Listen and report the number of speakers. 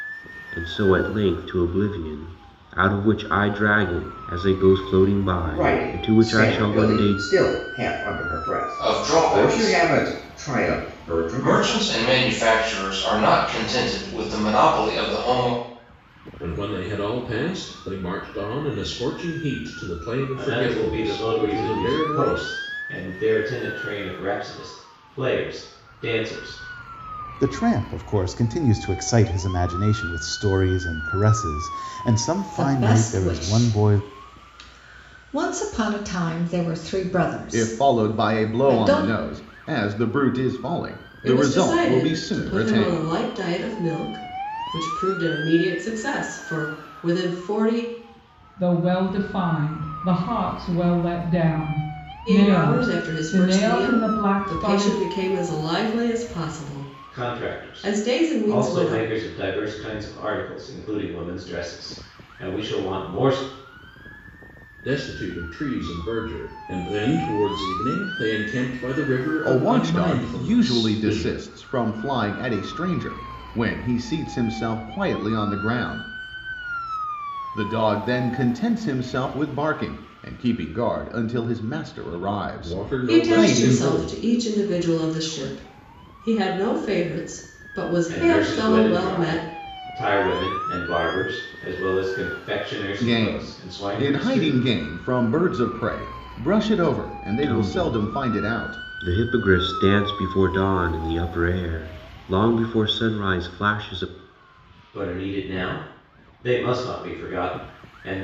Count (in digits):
10